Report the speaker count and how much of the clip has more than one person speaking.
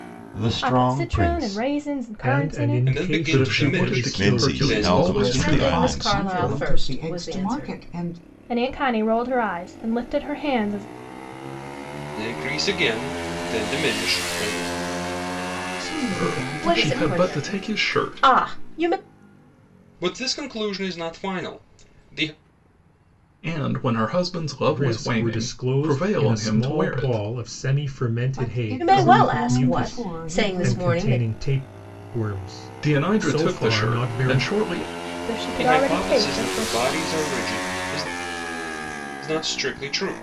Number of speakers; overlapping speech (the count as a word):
nine, about 43%